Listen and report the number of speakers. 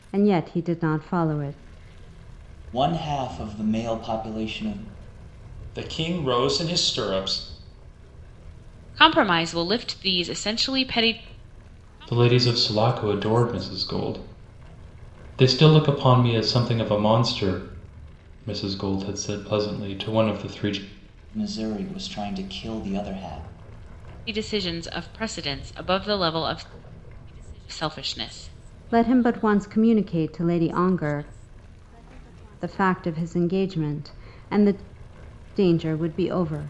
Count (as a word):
five